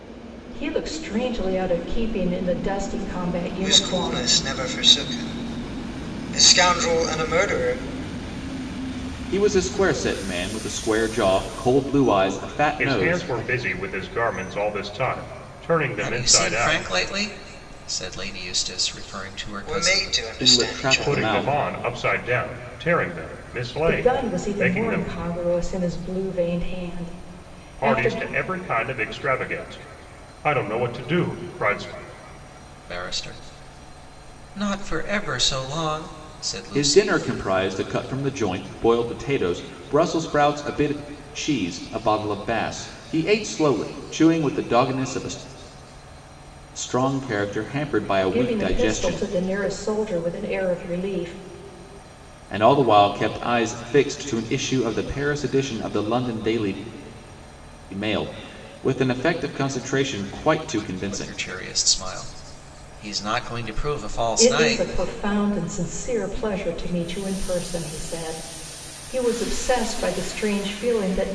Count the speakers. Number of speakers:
5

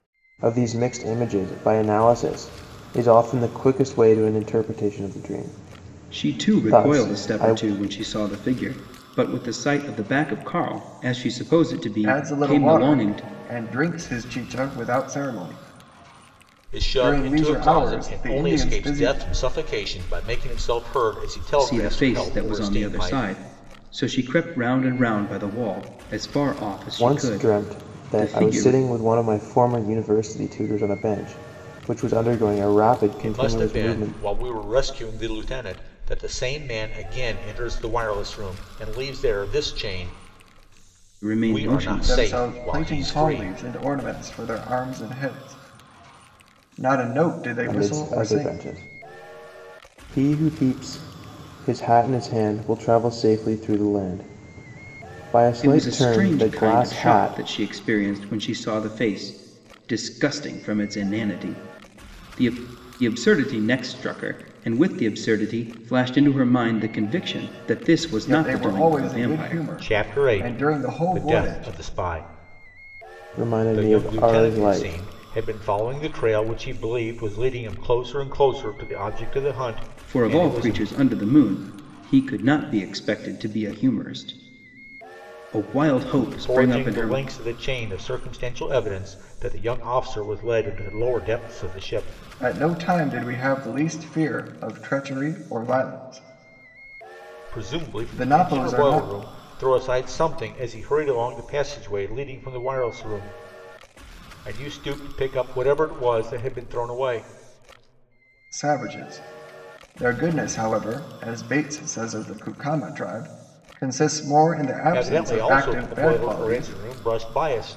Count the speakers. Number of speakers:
4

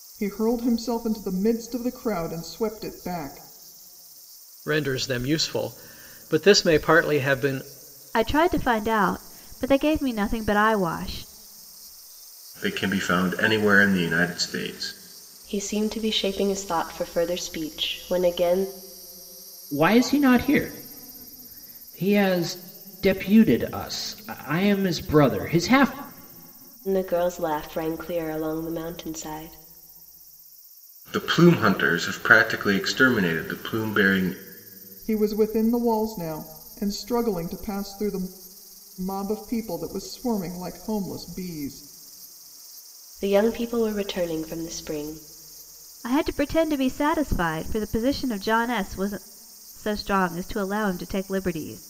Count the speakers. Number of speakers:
6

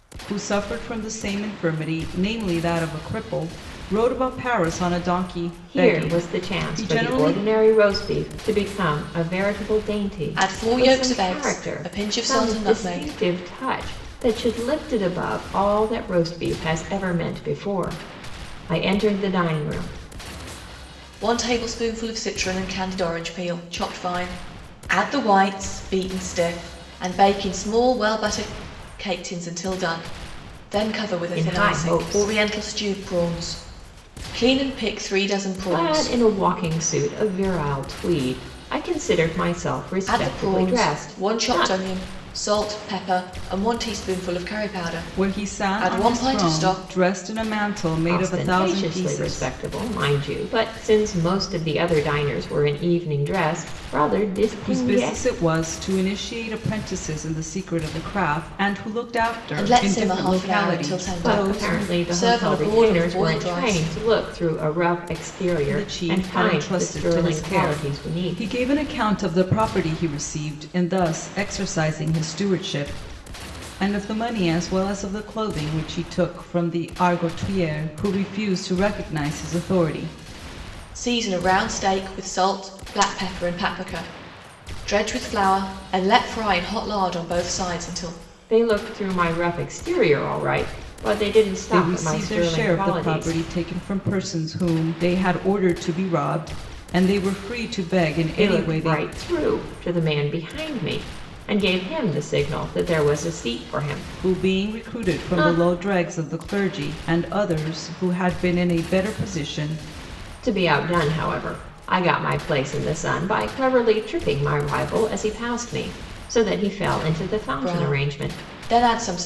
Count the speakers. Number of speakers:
3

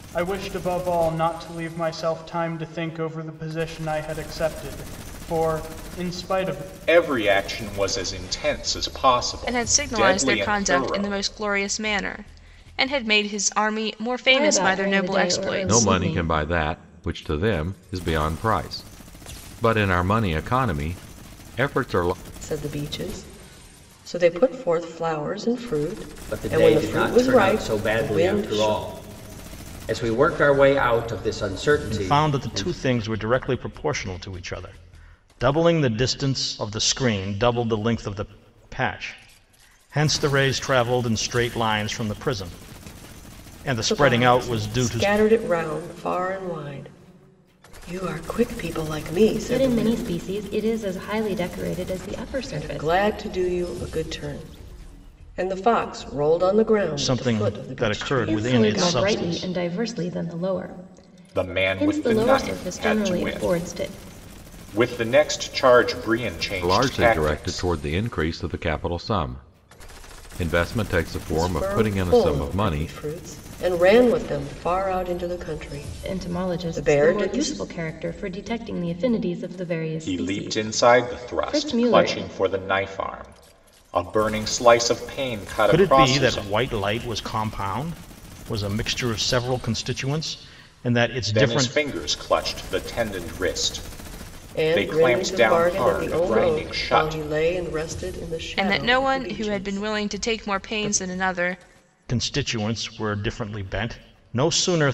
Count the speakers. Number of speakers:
8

